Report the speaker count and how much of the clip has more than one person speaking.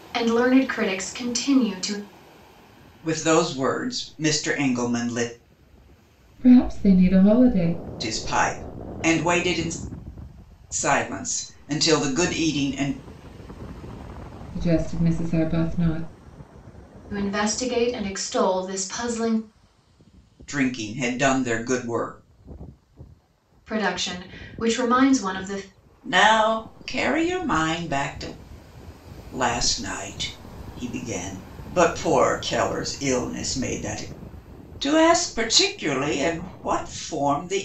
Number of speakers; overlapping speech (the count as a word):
three, no overlap